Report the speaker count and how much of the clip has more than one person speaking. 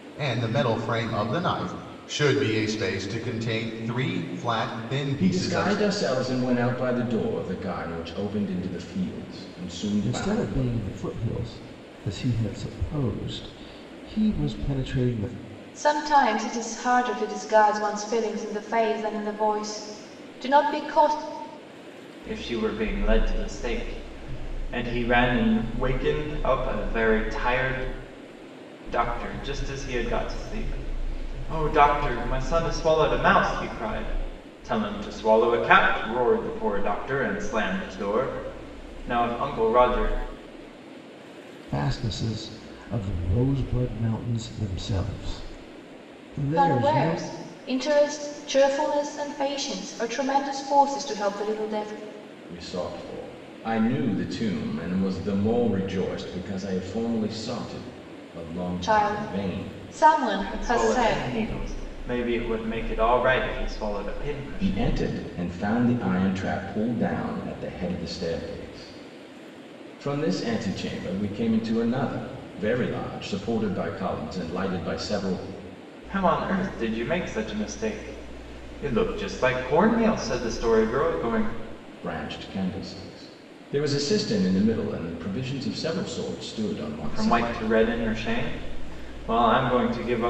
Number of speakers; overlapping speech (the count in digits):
5, about 5%